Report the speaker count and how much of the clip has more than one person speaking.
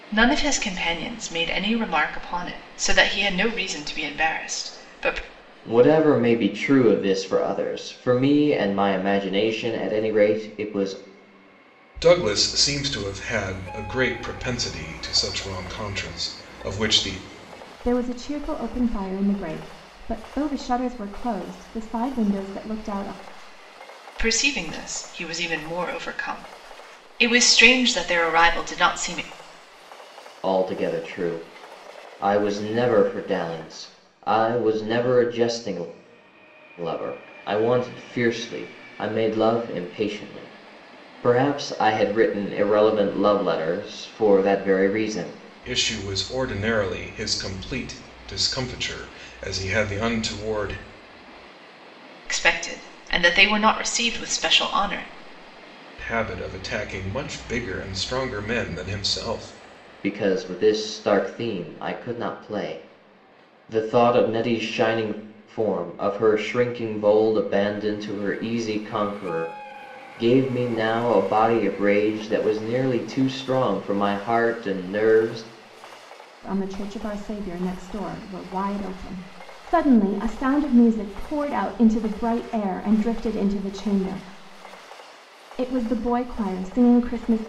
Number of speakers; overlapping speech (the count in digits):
4, no overlap